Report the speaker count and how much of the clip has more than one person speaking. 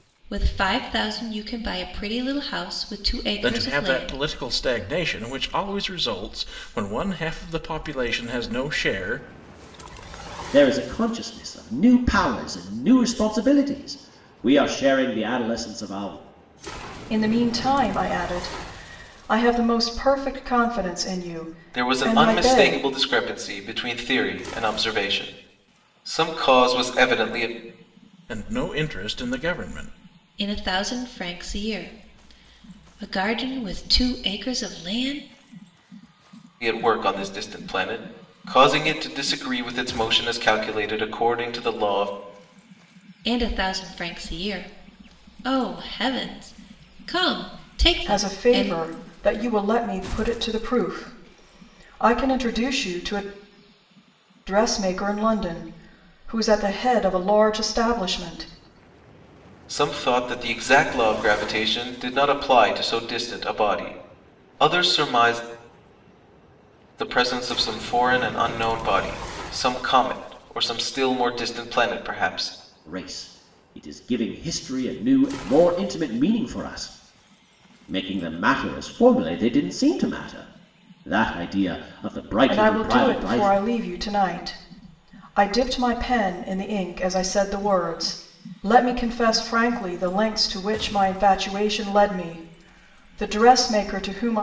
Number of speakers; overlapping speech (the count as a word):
five, about 4%